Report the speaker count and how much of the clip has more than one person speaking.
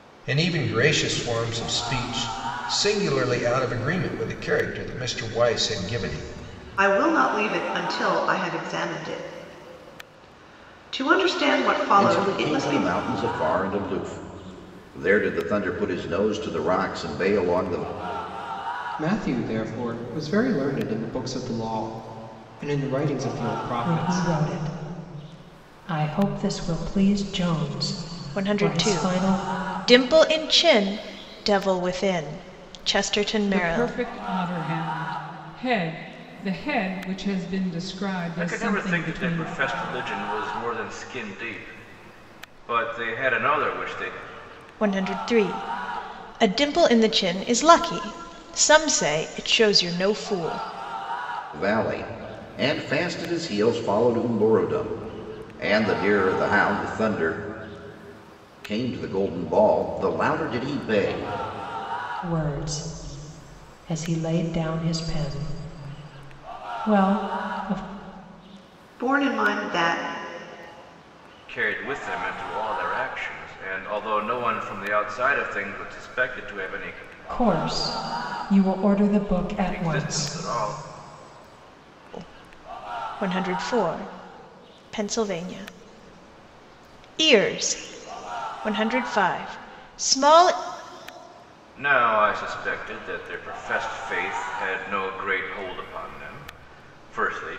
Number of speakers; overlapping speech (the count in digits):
8, about 5%